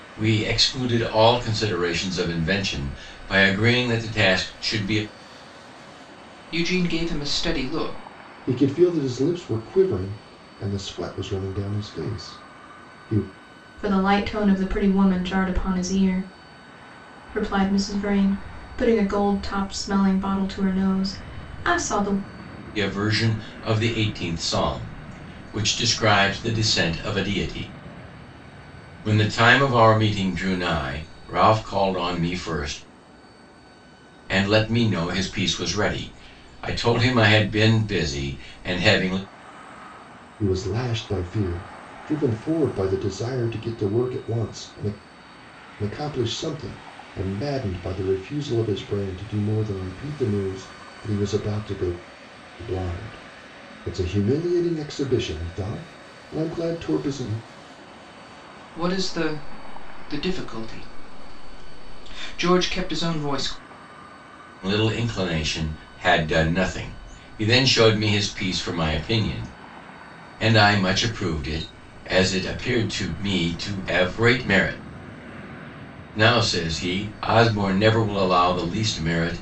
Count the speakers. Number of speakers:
4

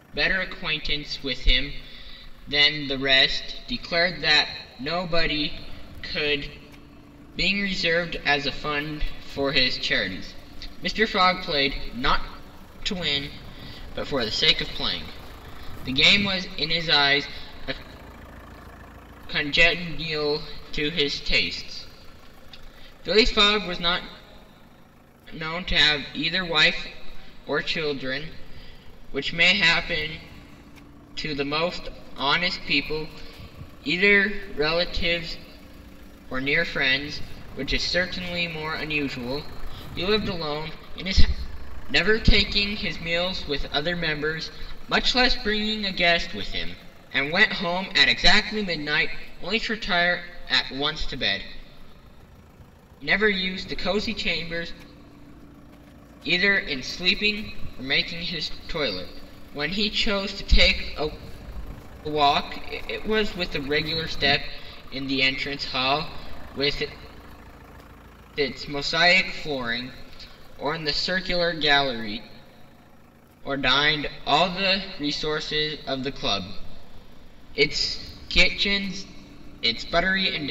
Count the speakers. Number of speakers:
1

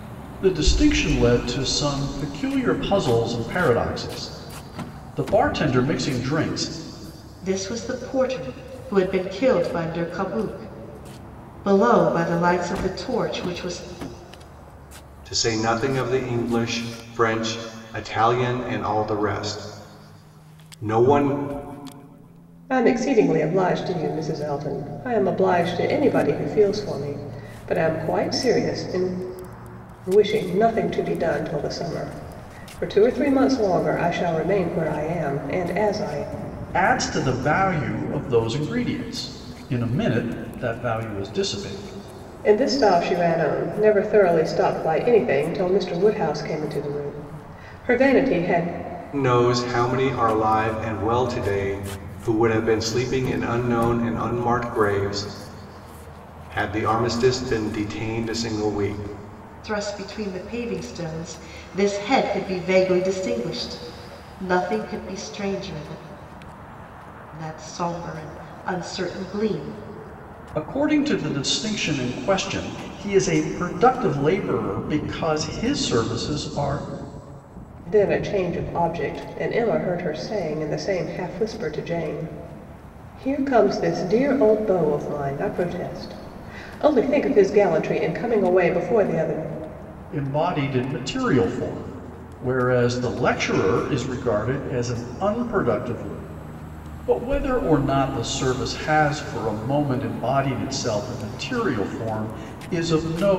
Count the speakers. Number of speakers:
4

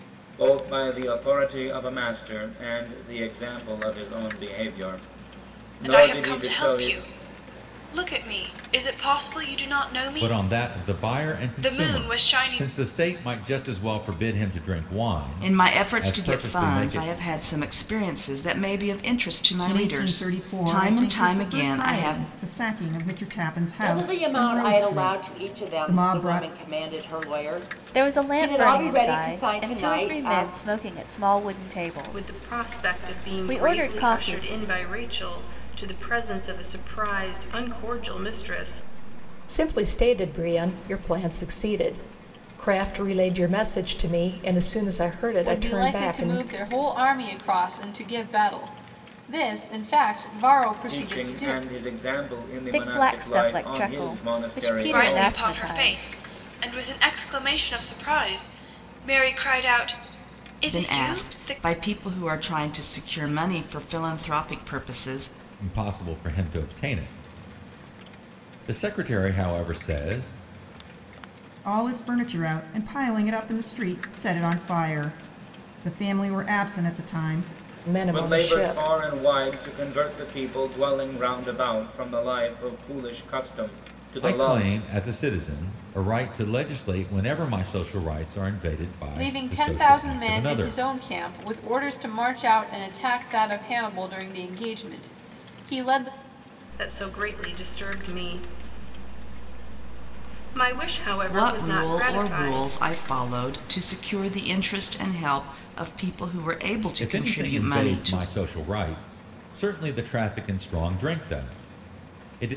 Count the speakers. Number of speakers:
10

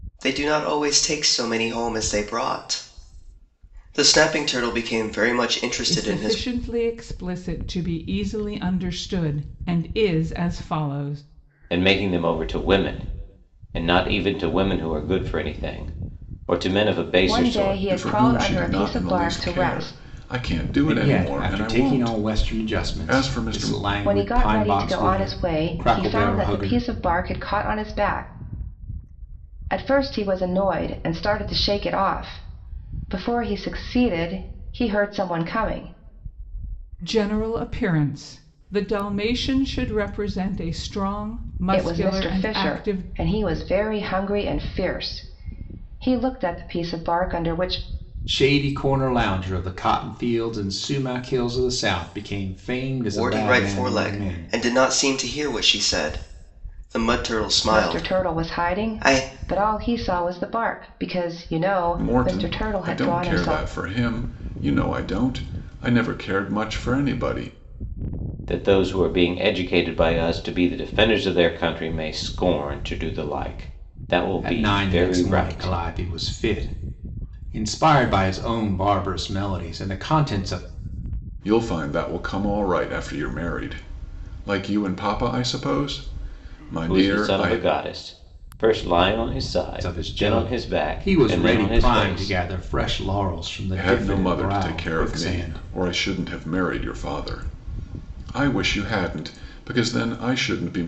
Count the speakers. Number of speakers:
6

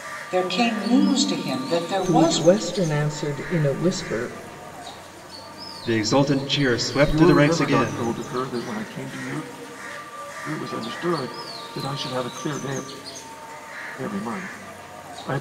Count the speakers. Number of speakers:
4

